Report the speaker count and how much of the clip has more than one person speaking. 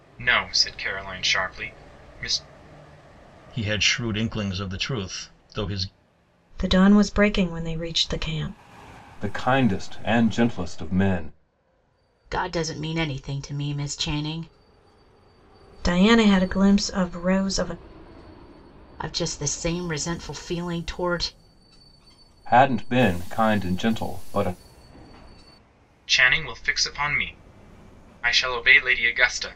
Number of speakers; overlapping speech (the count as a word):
five, no overlap